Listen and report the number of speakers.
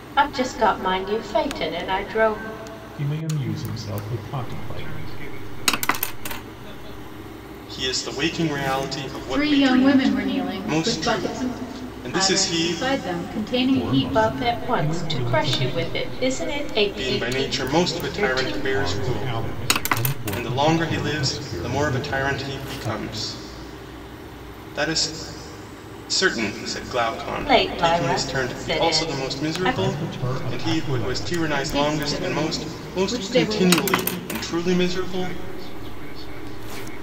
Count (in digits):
5